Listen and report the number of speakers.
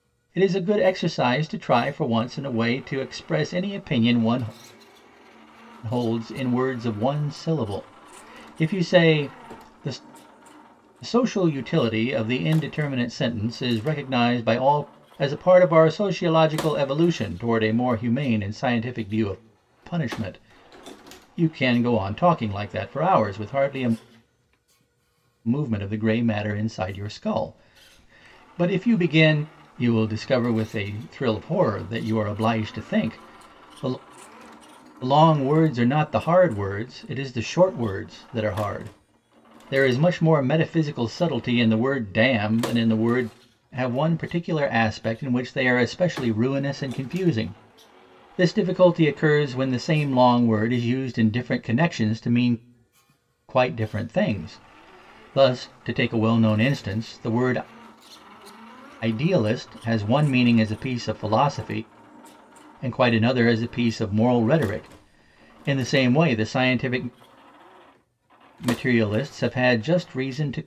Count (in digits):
1